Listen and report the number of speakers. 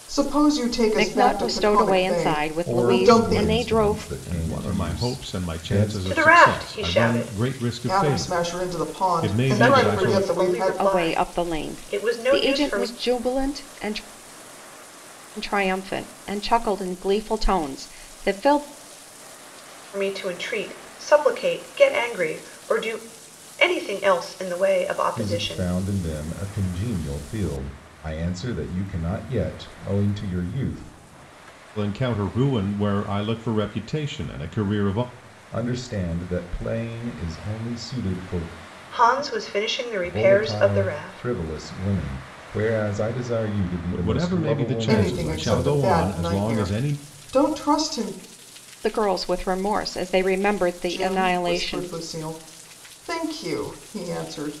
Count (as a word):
five